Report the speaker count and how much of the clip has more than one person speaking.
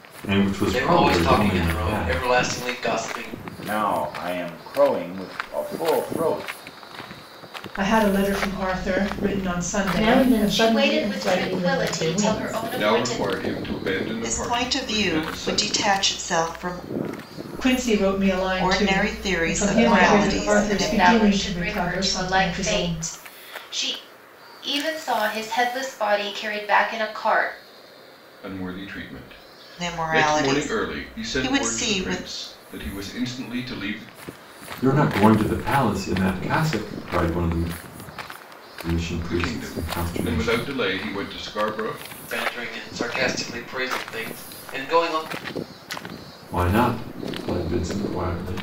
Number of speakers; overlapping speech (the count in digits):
8, about 31%